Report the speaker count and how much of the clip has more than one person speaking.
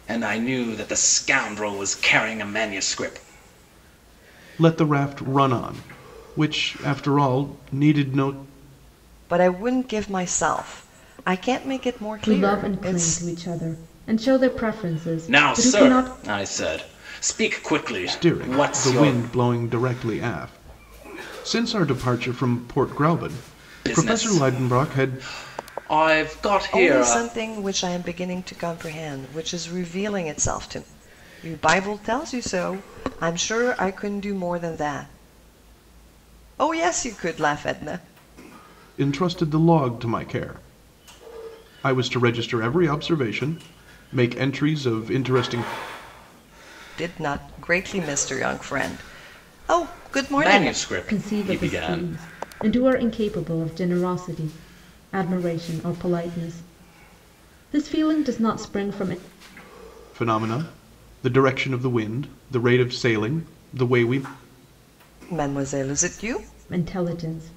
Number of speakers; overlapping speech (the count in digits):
4, about 9%